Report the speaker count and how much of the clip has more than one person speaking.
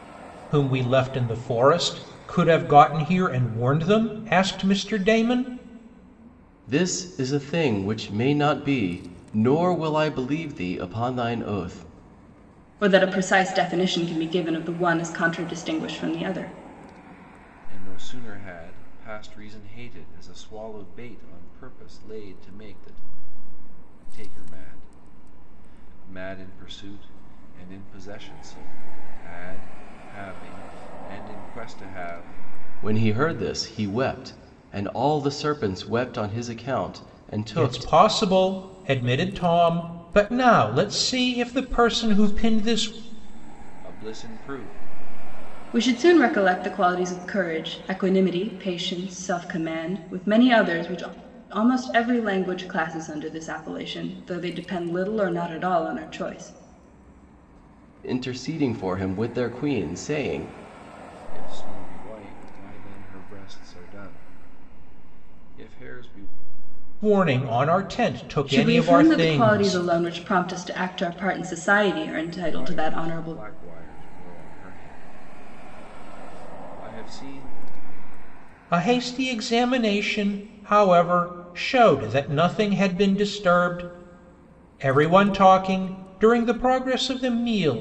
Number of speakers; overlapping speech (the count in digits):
4, about 4%